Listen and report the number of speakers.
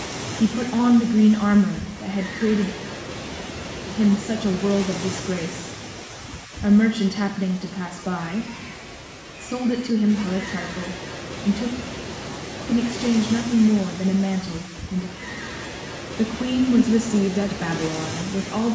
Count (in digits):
1